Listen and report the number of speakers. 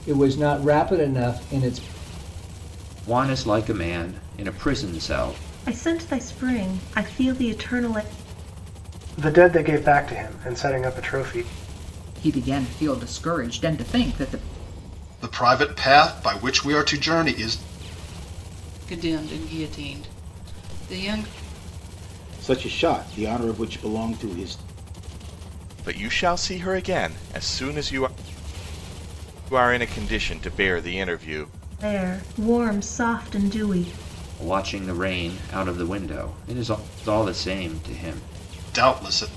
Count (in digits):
9